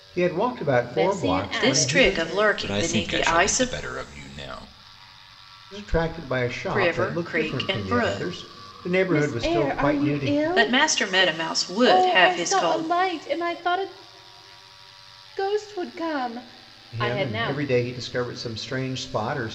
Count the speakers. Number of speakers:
four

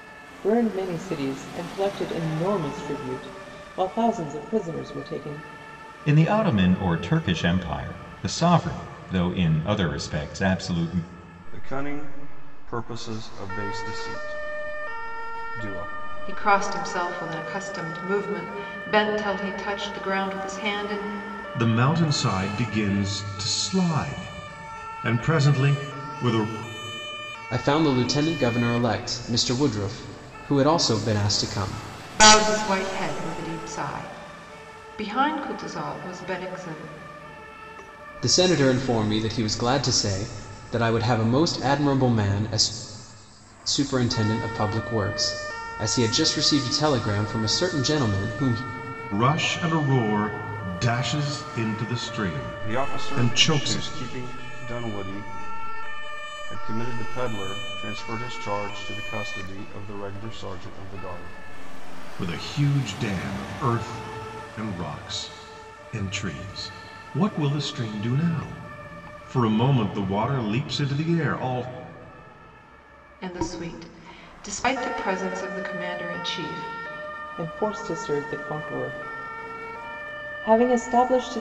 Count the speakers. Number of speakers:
six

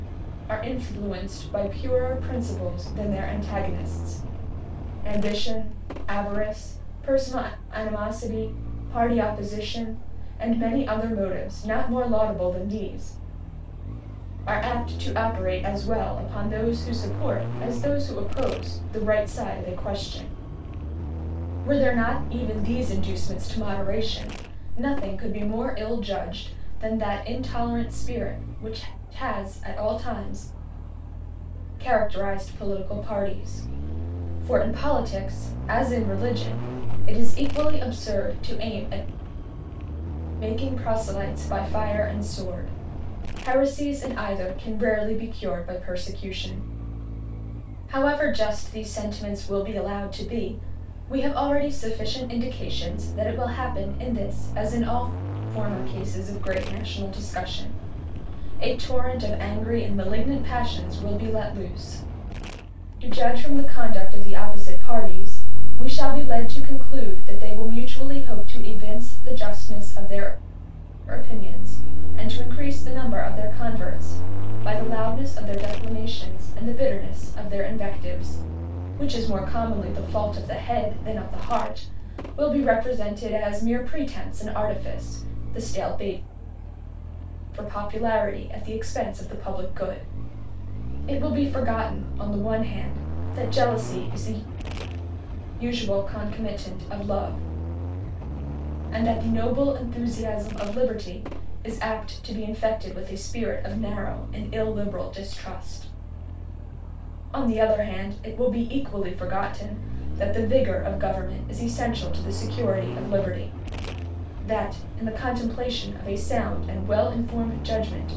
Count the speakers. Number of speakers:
one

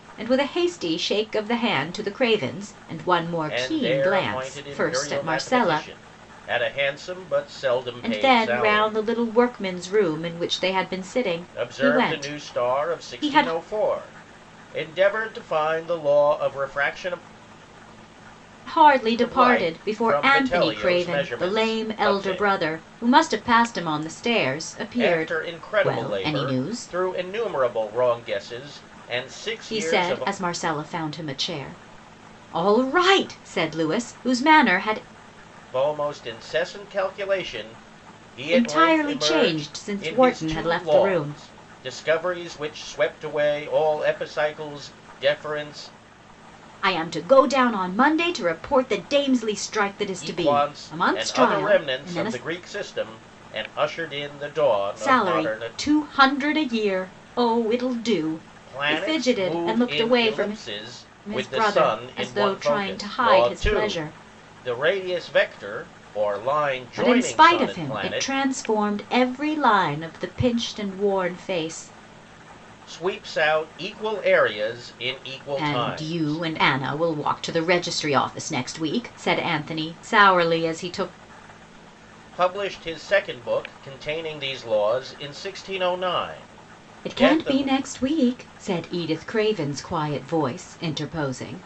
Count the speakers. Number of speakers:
two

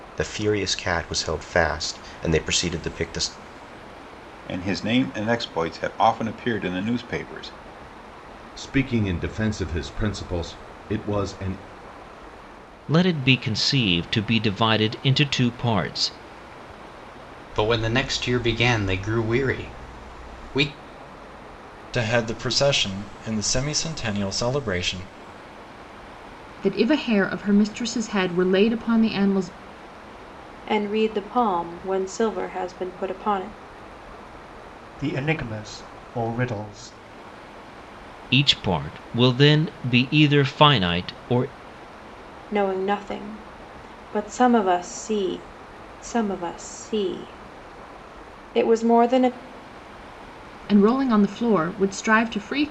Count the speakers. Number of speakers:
nine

